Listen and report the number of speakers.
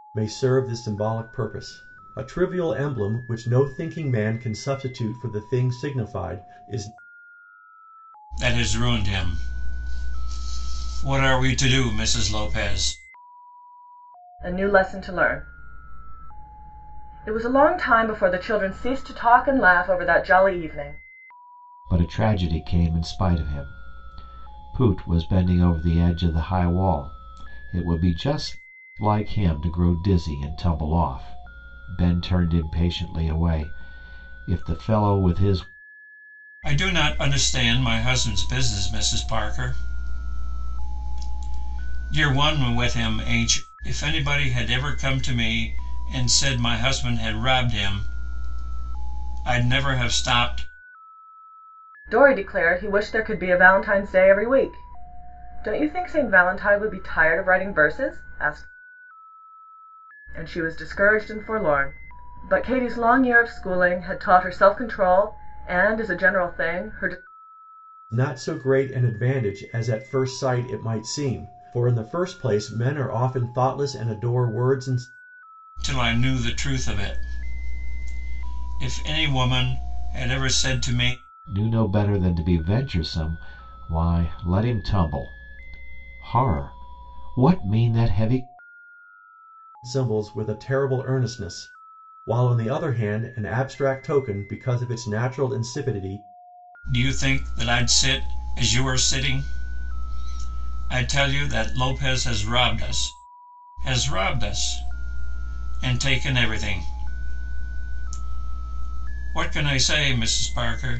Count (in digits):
4